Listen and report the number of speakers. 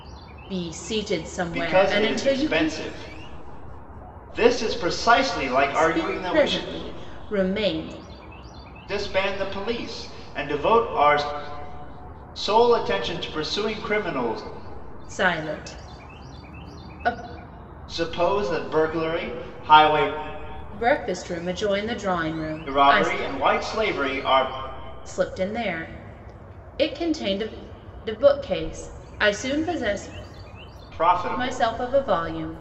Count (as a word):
two